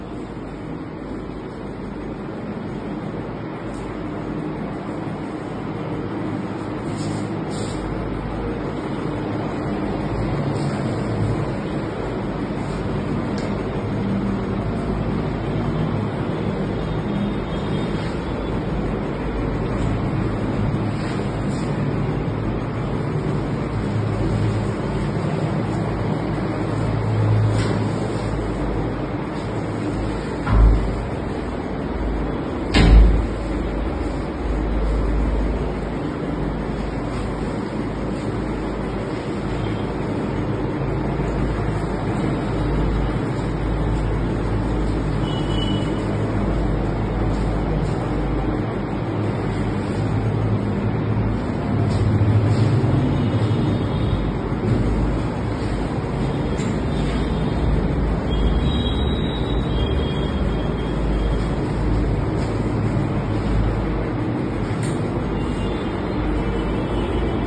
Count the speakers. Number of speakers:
0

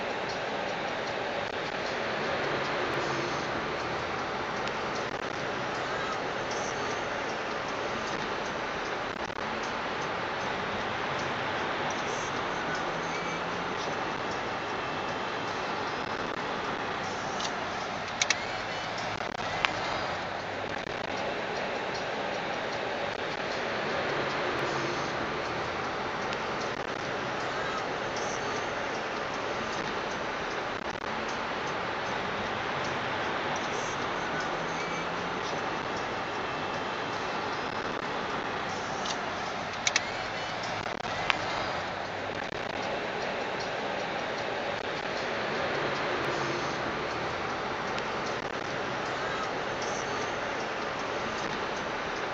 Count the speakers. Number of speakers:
0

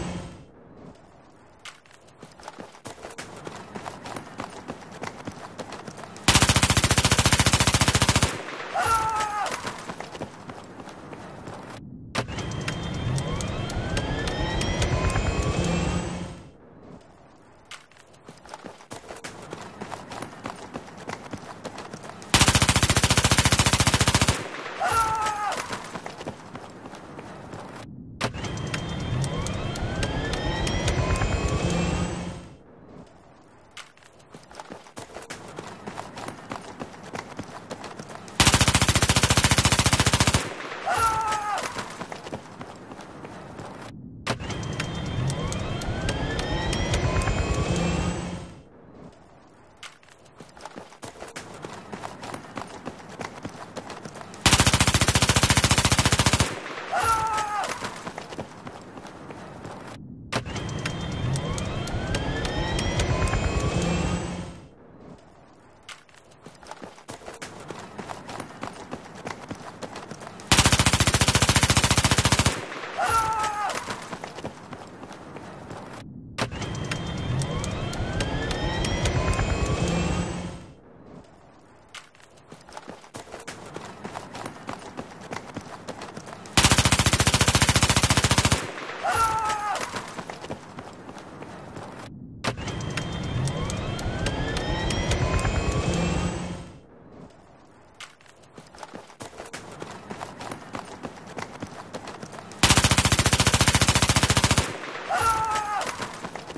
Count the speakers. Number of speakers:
0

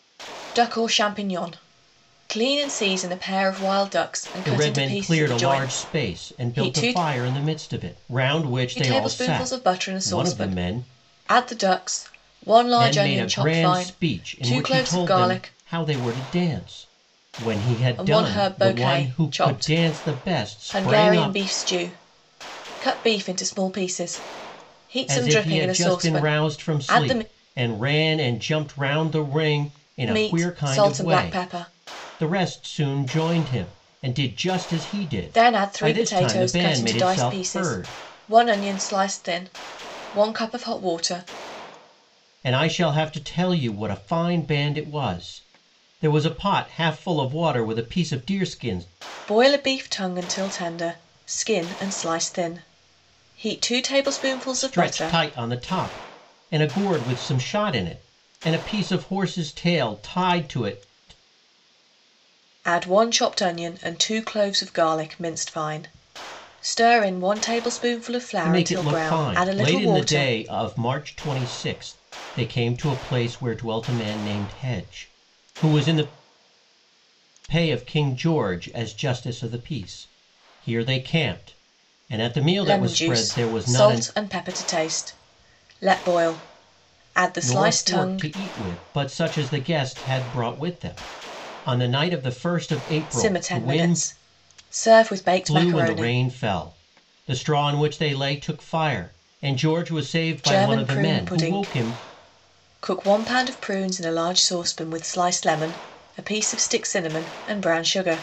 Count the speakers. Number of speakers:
2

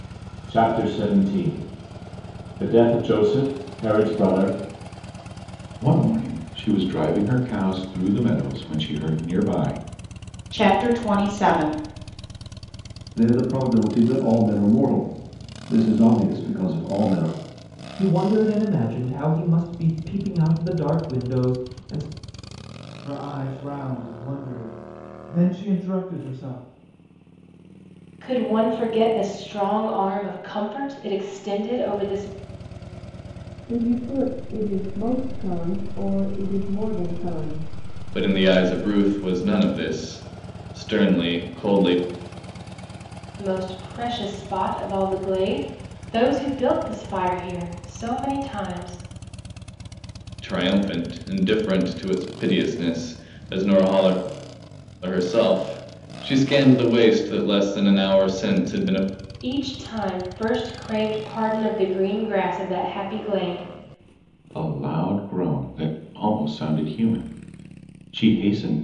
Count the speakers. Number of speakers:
9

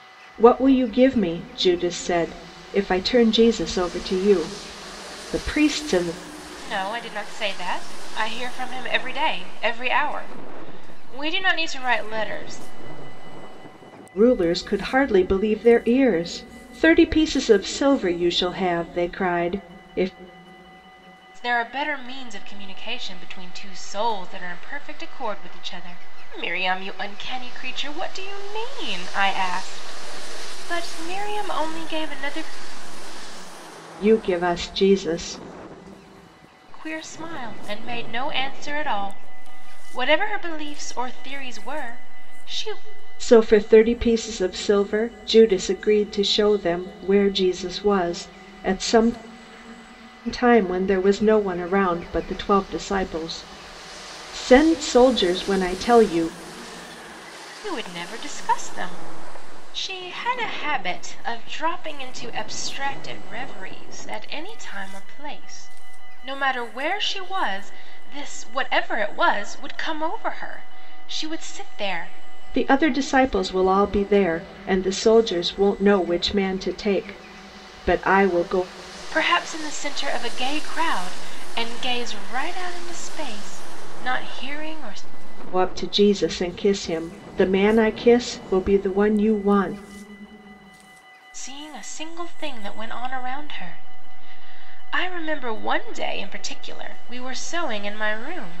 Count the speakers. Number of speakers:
2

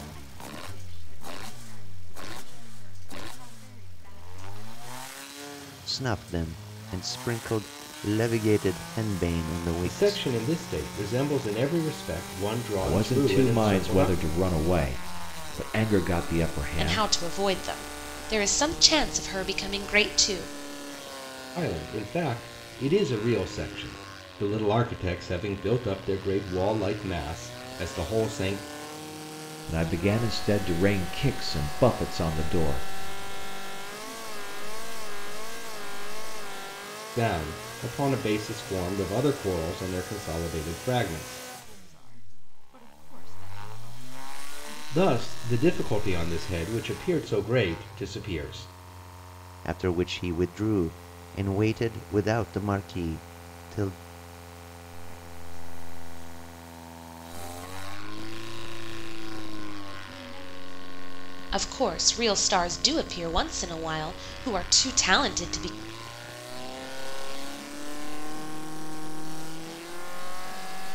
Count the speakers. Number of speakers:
5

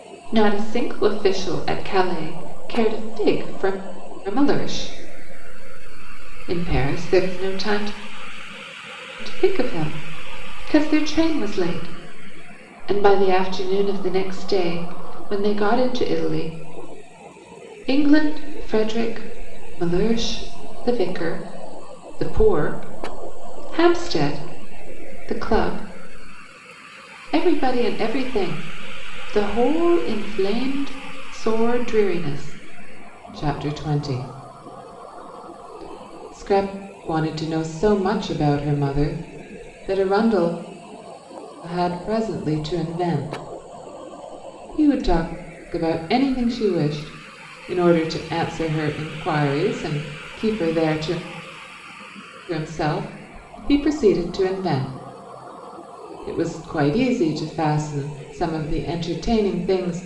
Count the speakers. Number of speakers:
1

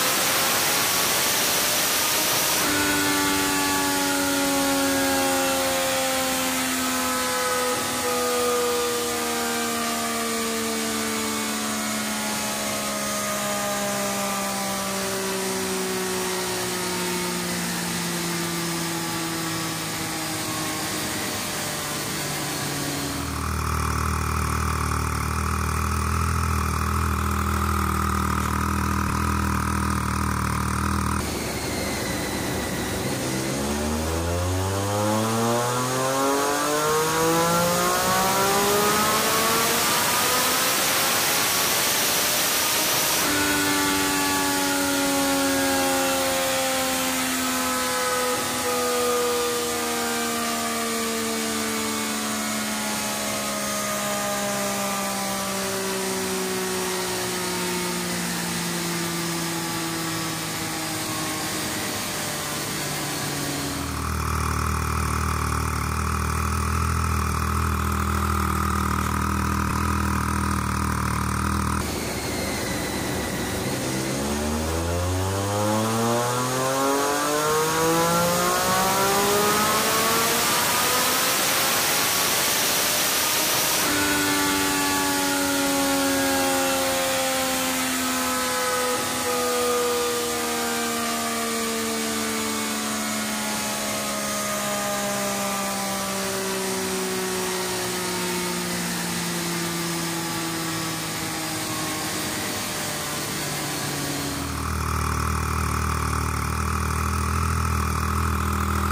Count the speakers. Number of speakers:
0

